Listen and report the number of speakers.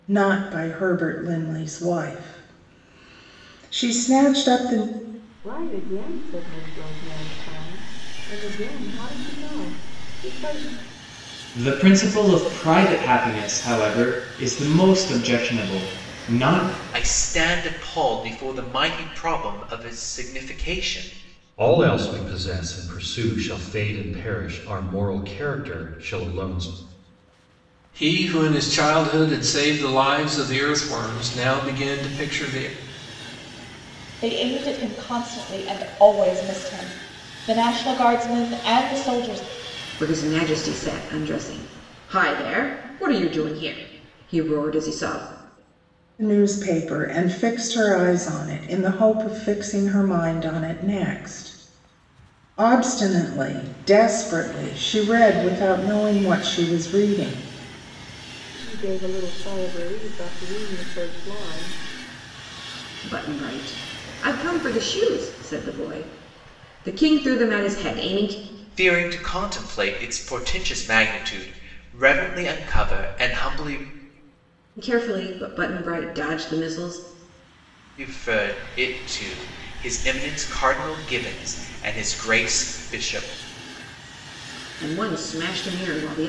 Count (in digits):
8